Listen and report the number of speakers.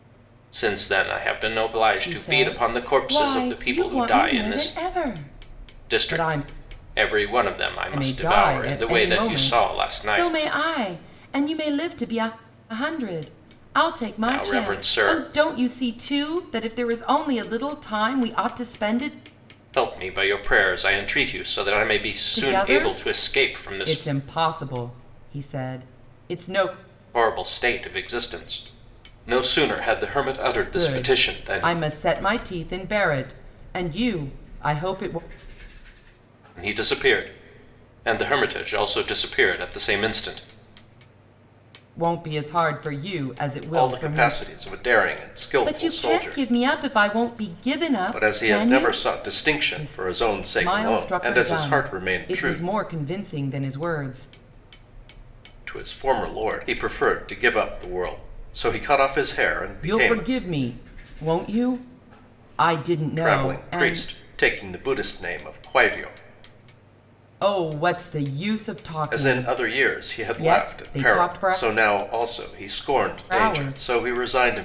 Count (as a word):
two